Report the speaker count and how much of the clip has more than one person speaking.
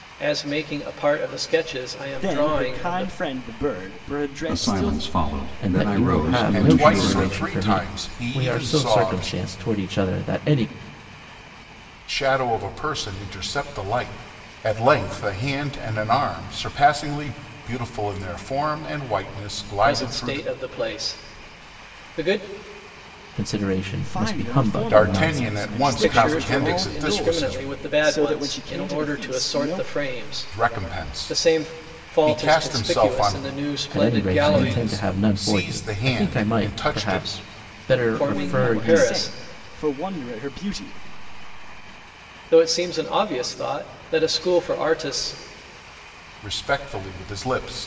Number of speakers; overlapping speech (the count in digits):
5, about 39%